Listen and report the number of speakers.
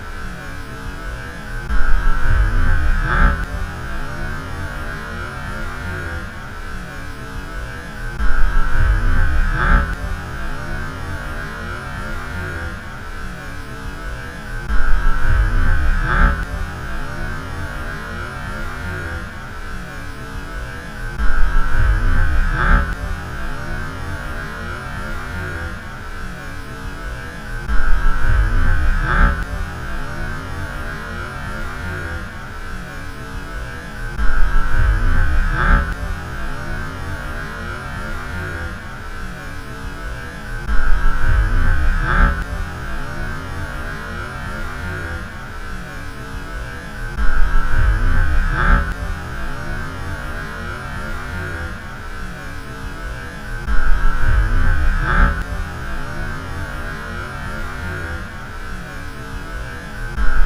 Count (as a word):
zero